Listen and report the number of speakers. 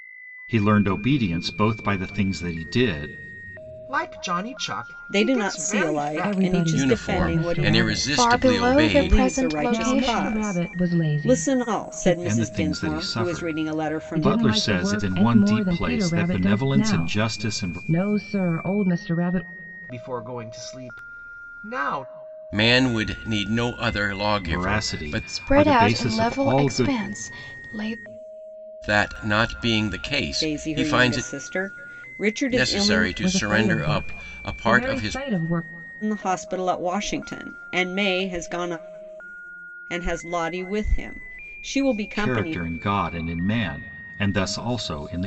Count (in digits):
6